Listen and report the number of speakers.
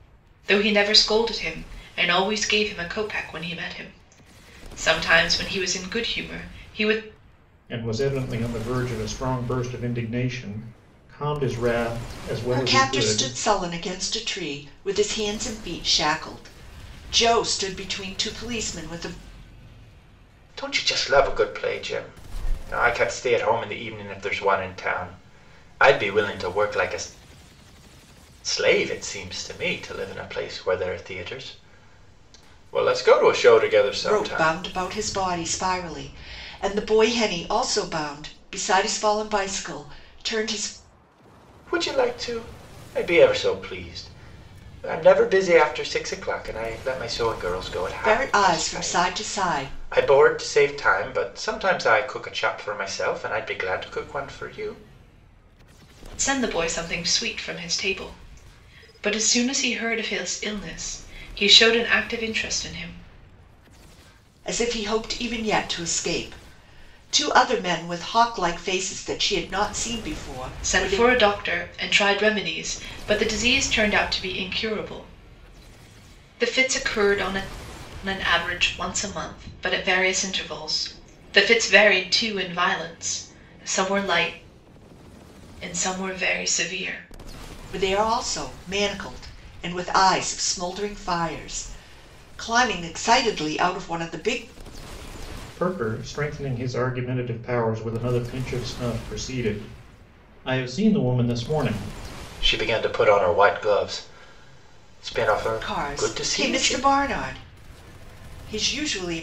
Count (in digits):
4